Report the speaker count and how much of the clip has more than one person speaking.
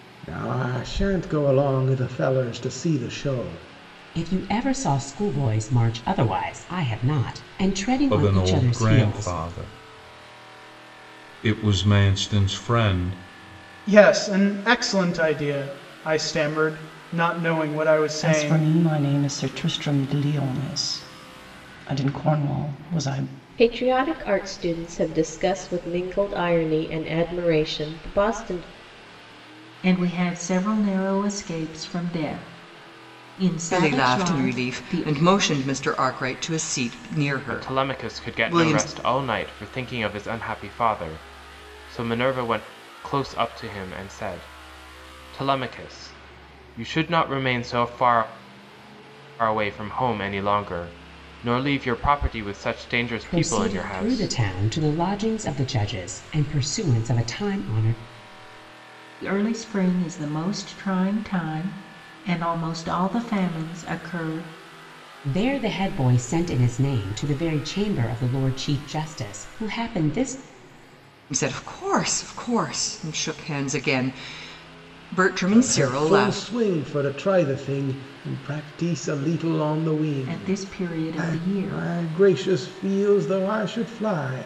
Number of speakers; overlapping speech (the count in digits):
9, about 9%